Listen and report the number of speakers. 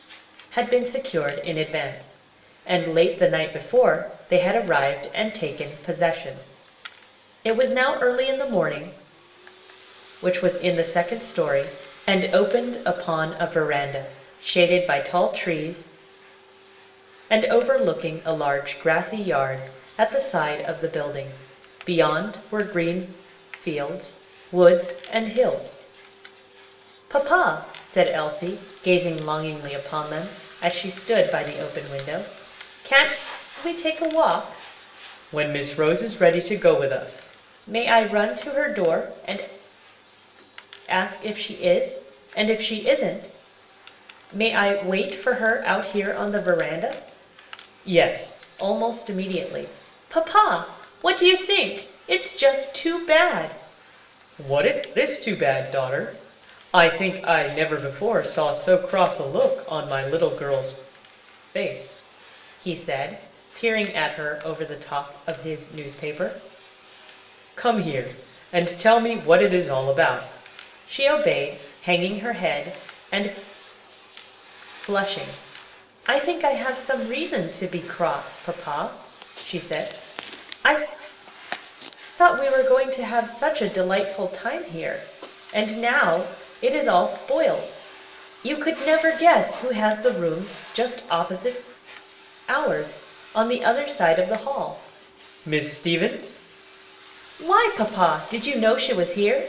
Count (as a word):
one